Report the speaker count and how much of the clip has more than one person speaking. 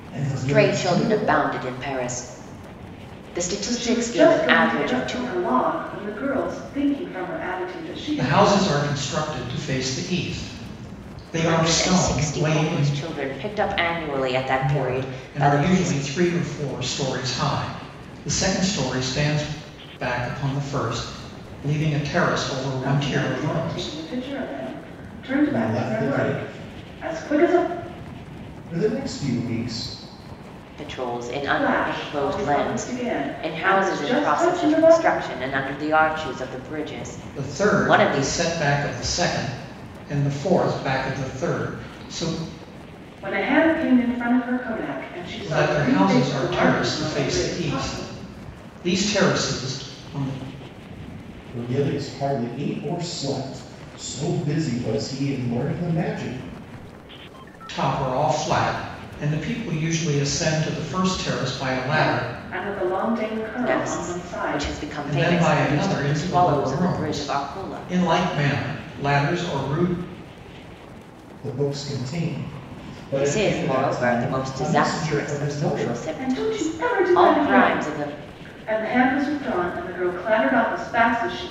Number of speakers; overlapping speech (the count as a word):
four, about 33%